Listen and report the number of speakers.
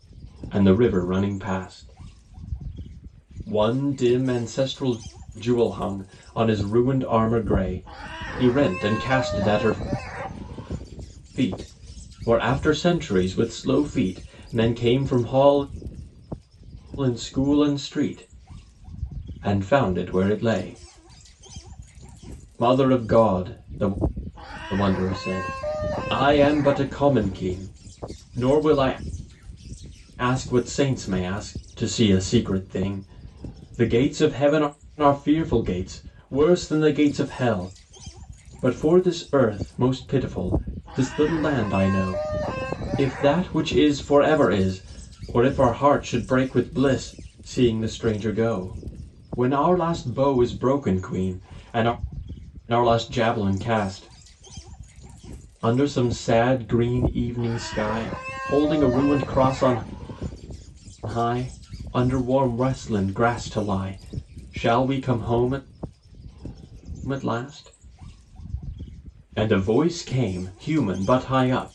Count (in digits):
1